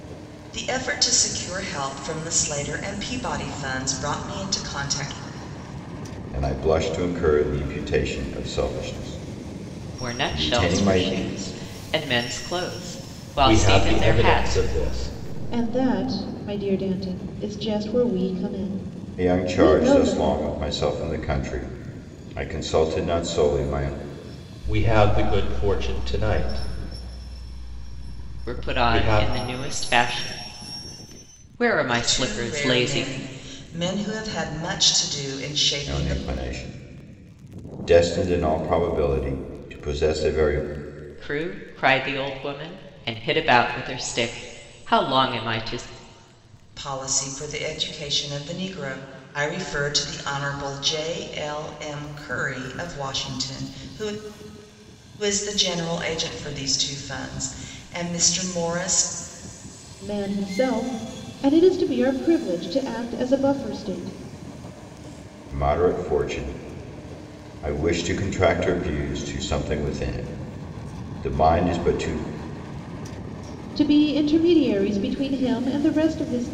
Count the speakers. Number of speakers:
5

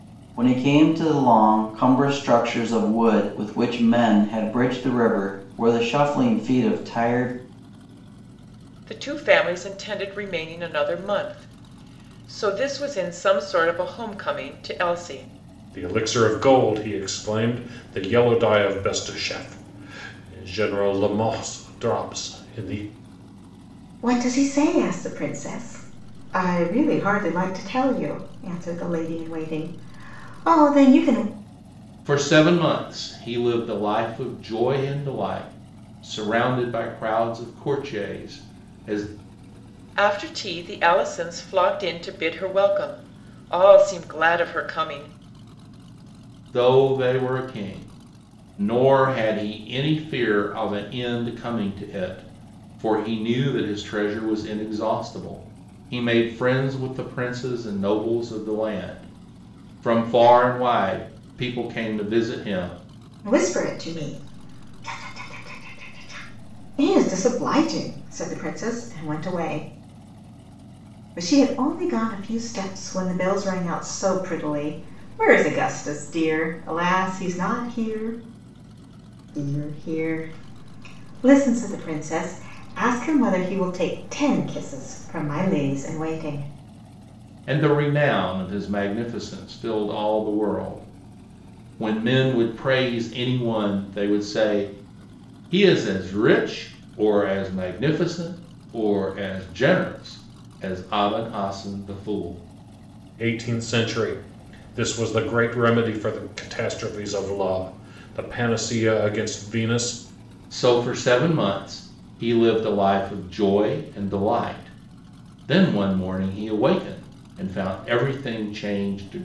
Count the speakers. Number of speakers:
5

